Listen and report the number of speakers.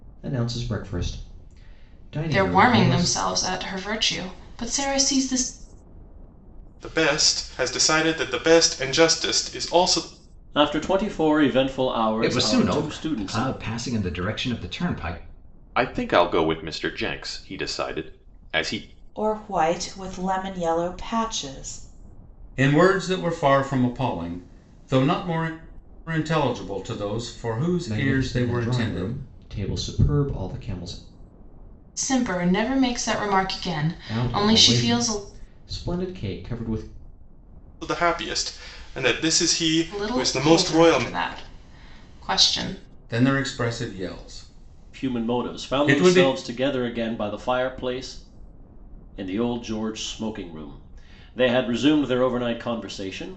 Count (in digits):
8